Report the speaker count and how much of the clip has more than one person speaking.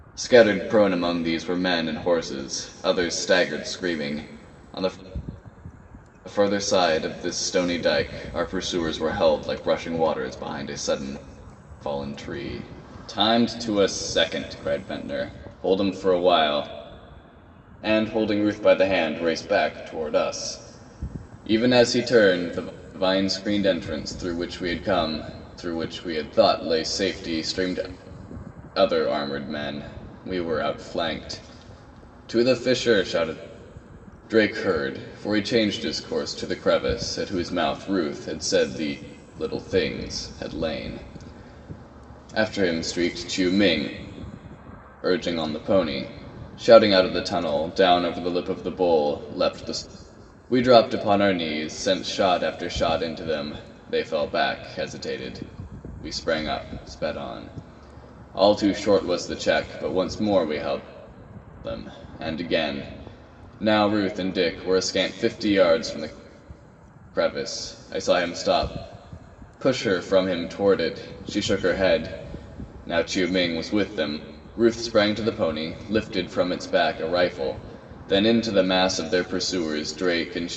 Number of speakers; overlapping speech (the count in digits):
1, no overlap